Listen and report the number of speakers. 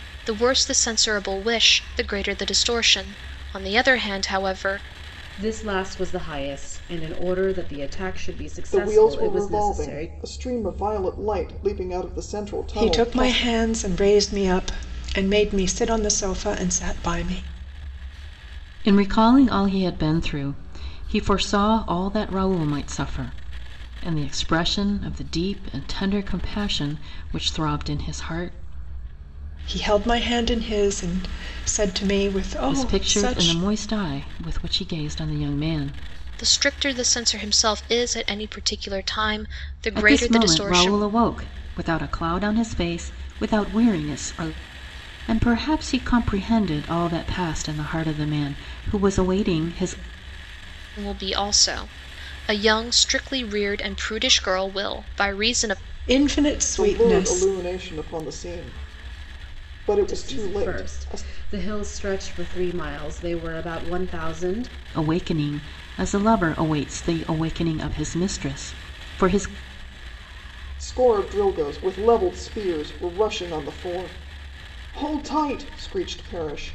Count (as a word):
five